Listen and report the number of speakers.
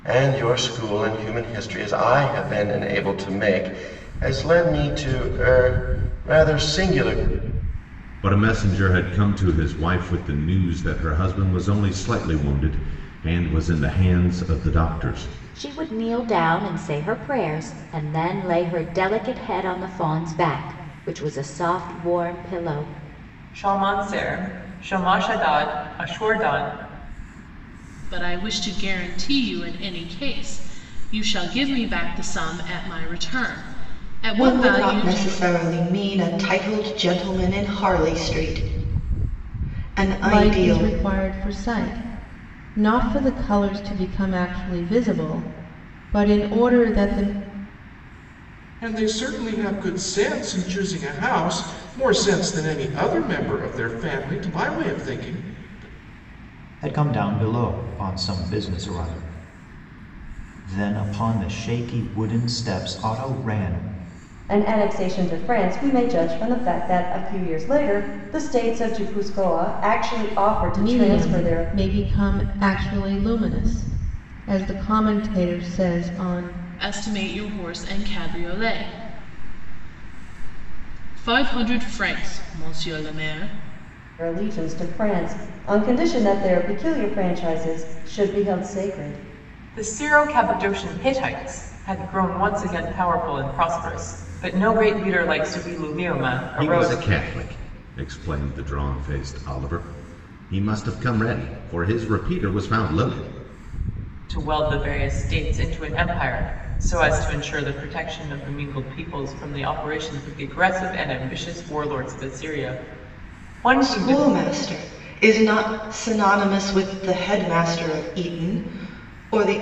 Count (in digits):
10